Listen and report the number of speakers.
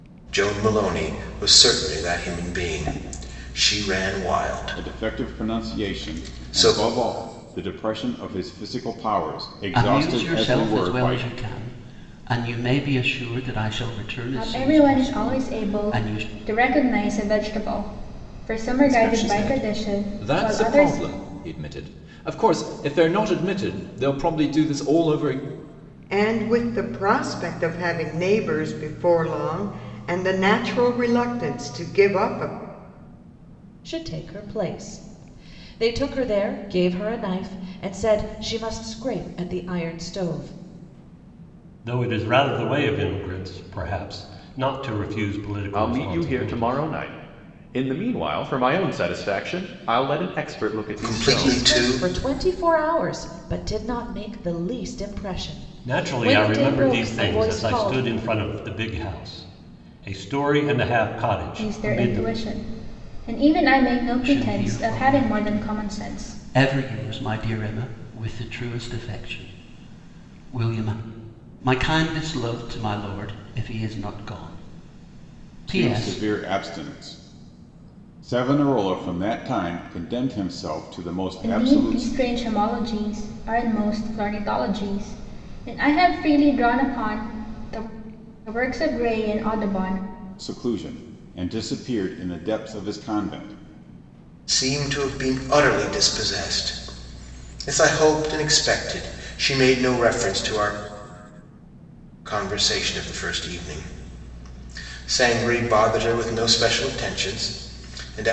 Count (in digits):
9